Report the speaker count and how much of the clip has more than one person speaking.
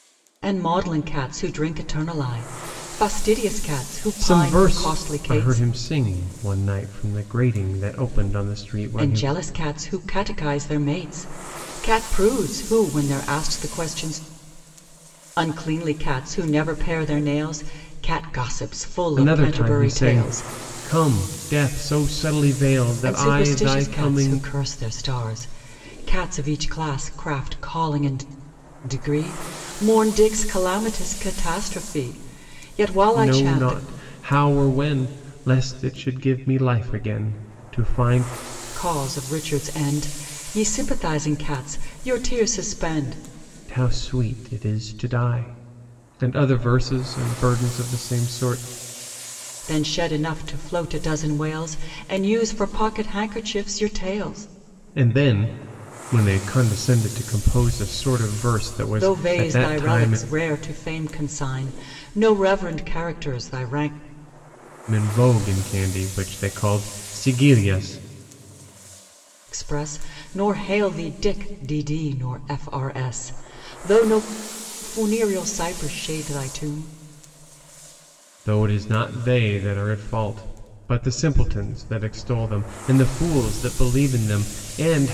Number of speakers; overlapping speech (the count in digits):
2, about 8%